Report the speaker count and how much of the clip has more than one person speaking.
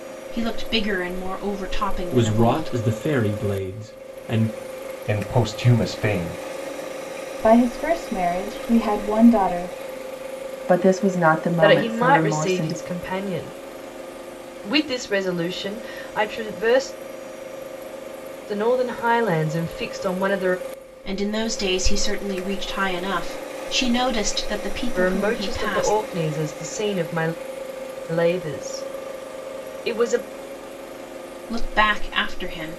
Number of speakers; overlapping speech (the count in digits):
6, about 9%